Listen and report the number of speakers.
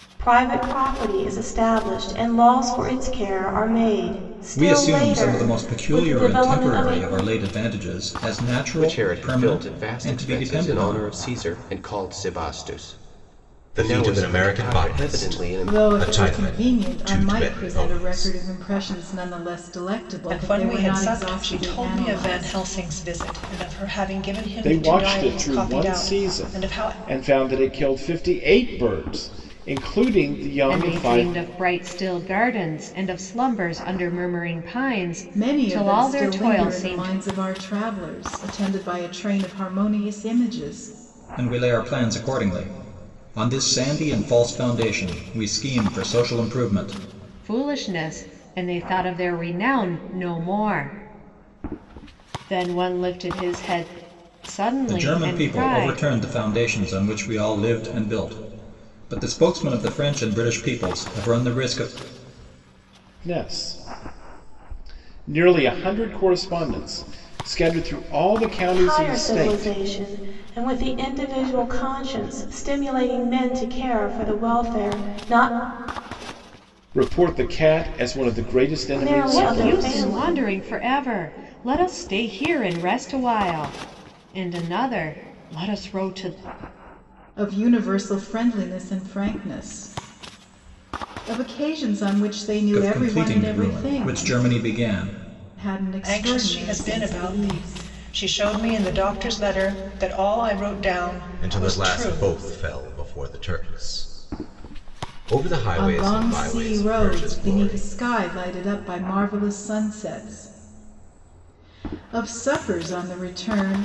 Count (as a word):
eight